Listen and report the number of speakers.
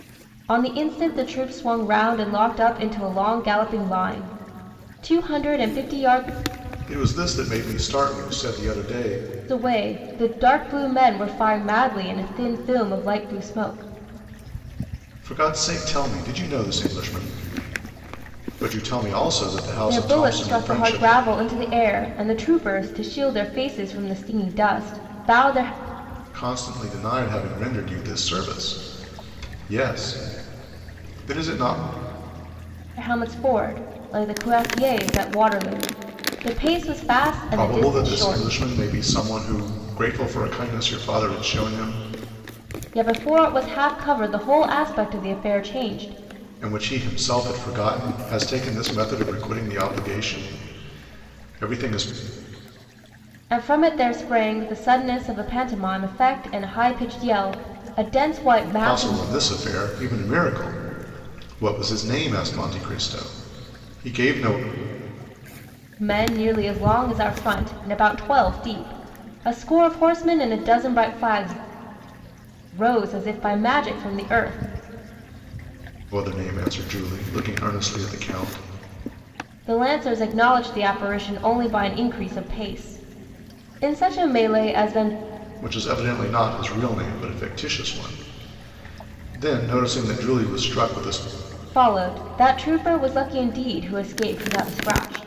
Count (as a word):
two